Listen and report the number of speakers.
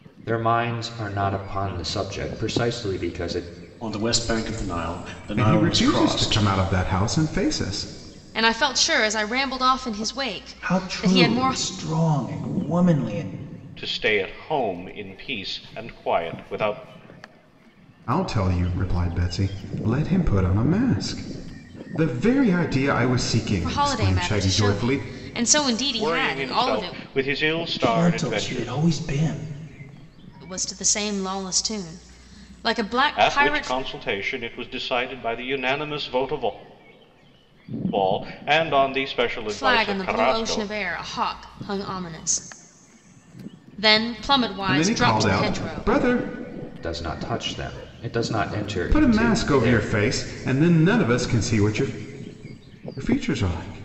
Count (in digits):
6